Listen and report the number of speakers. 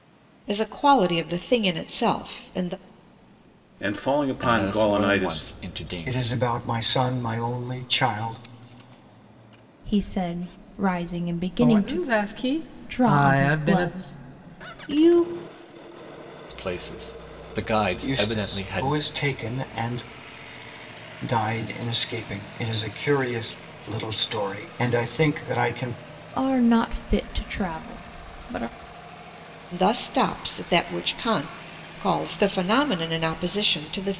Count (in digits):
6